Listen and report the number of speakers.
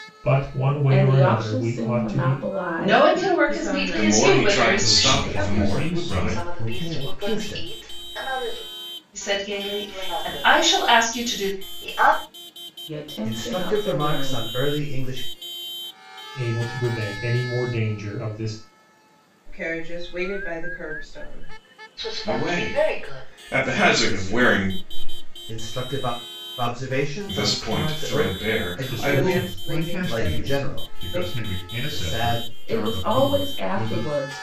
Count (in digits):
8